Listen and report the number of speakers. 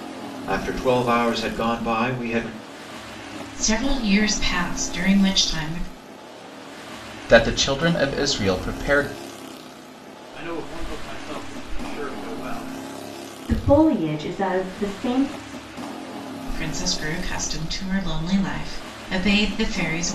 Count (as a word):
five